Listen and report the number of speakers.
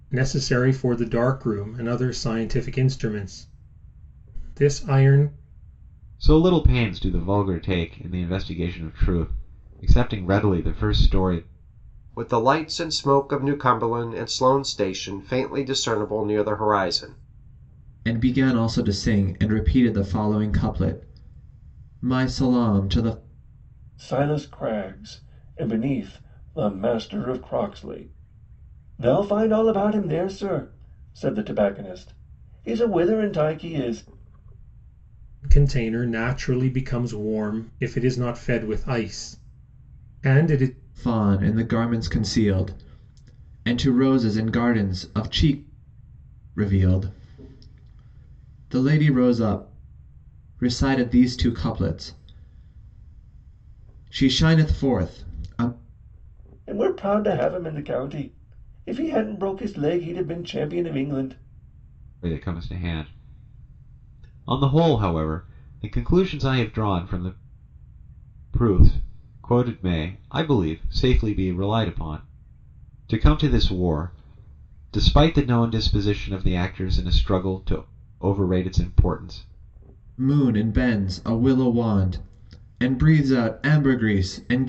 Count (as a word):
five